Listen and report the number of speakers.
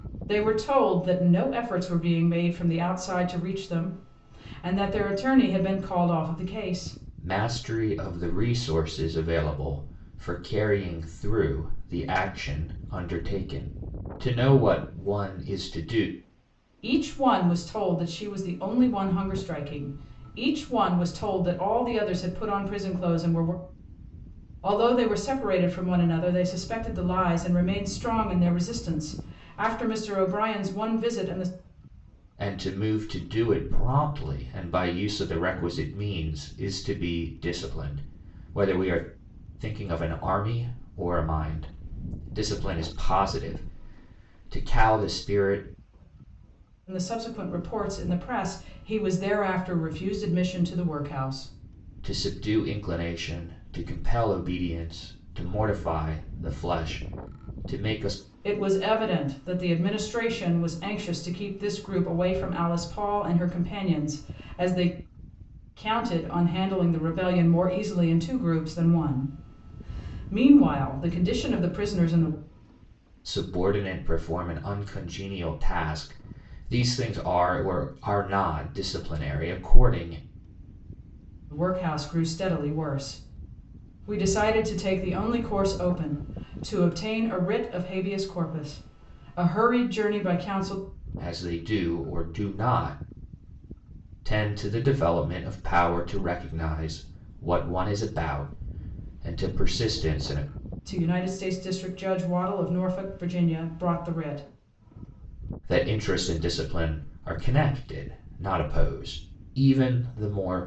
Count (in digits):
2